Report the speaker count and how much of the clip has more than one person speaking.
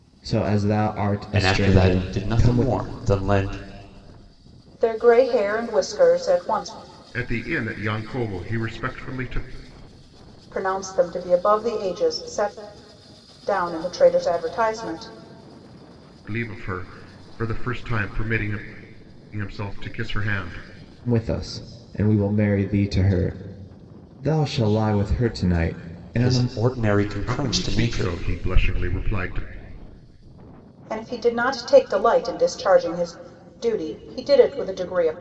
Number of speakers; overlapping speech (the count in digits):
4, about 8%